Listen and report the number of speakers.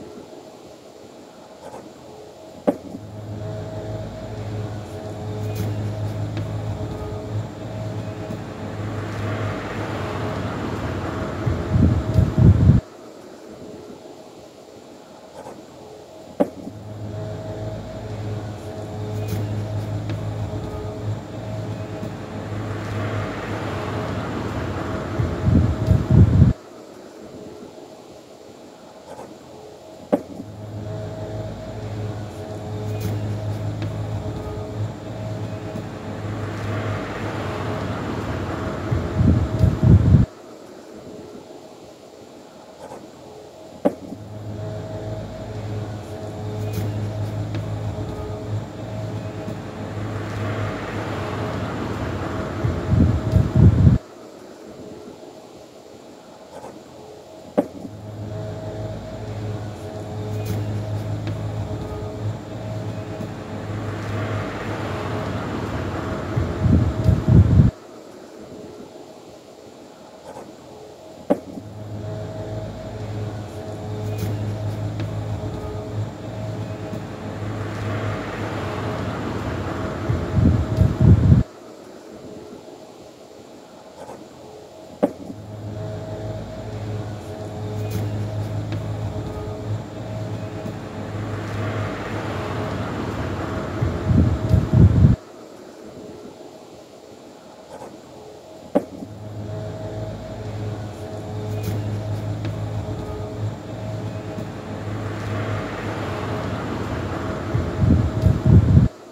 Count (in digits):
0